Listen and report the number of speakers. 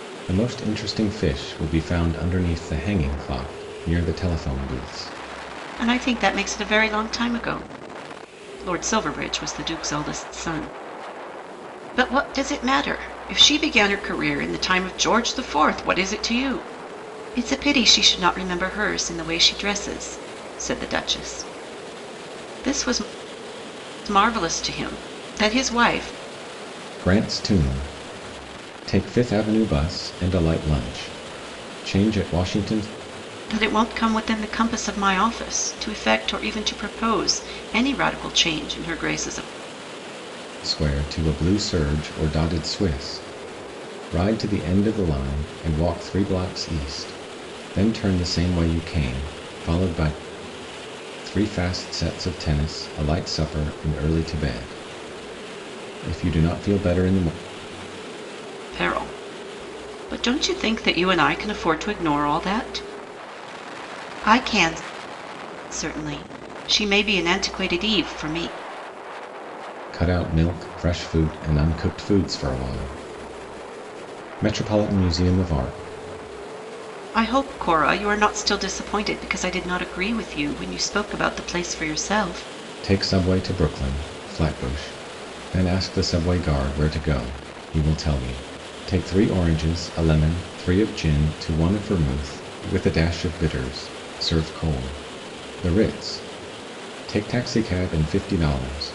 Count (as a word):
two